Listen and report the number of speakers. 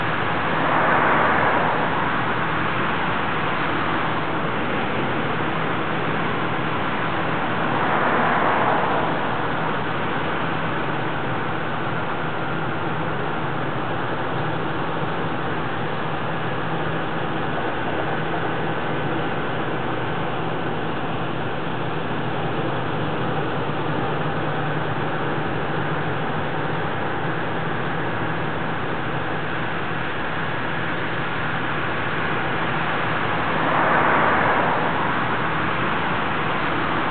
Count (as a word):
zero